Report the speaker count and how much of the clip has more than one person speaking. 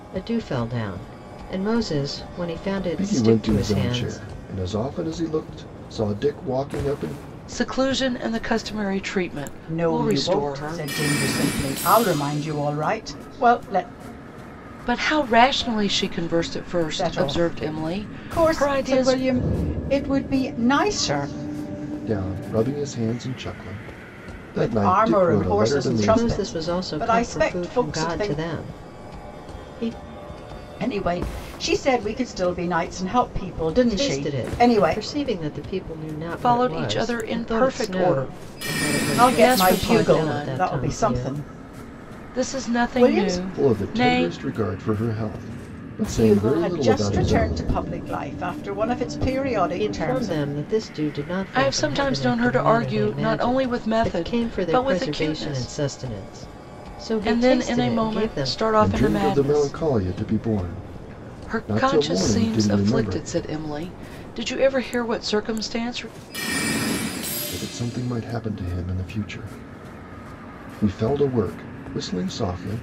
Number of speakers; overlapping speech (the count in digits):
4, about 40%